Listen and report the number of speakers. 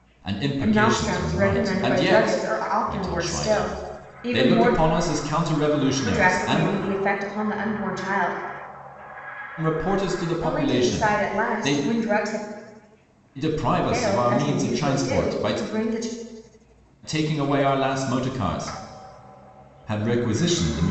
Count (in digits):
2